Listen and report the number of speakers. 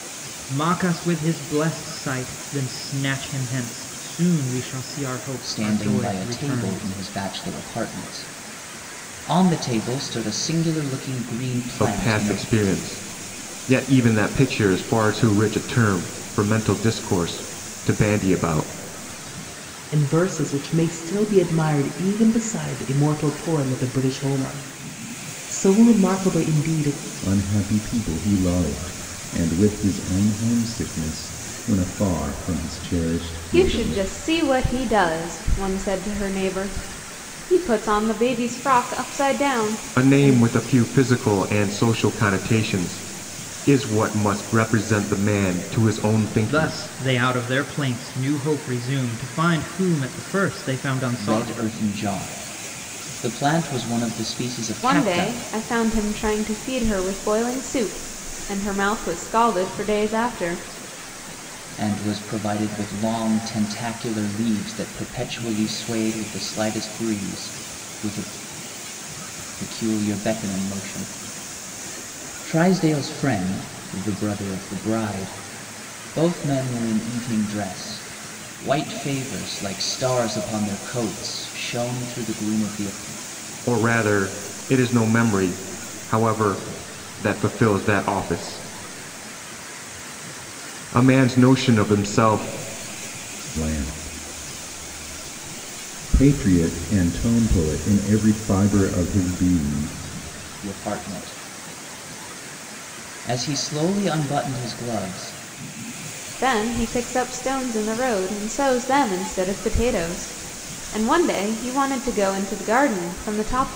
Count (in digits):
6